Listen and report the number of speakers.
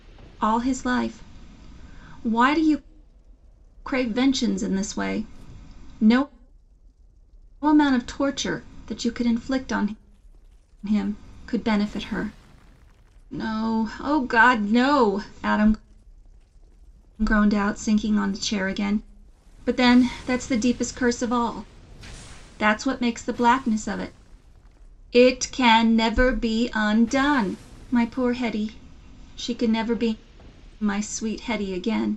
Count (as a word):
one